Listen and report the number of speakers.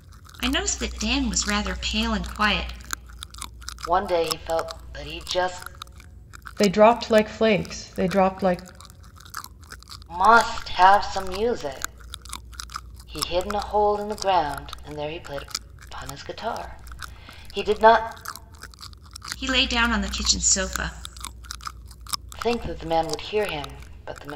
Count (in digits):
3